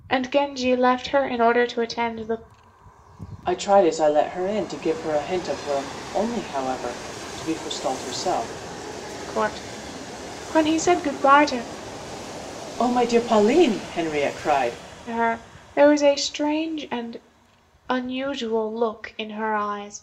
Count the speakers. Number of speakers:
2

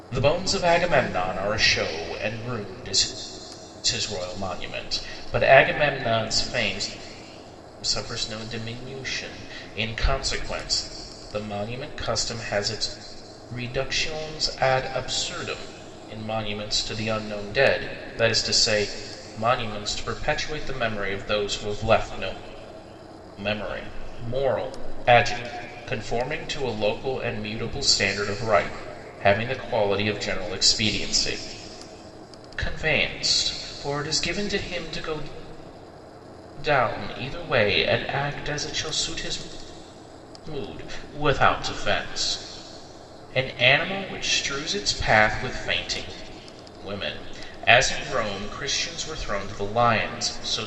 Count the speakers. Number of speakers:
1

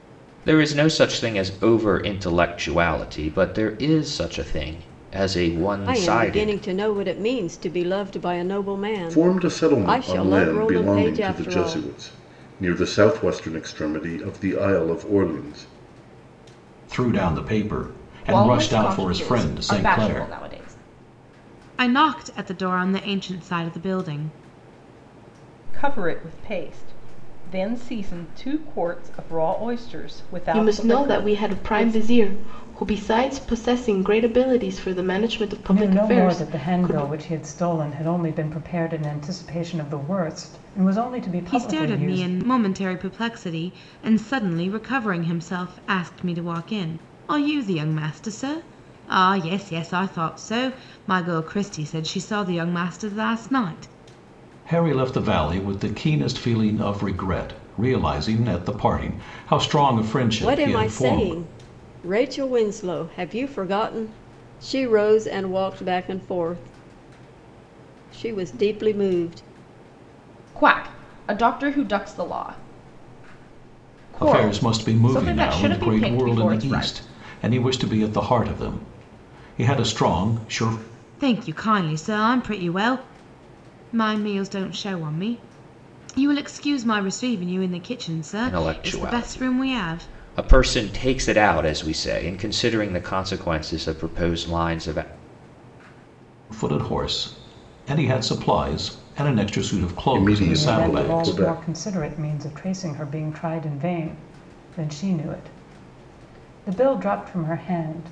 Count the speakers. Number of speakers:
9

